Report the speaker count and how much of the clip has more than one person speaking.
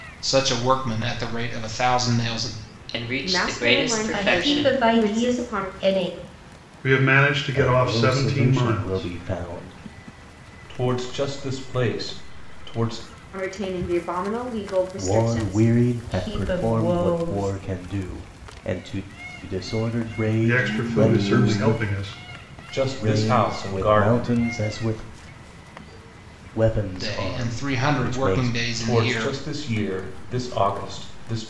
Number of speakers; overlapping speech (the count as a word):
seven, about 36%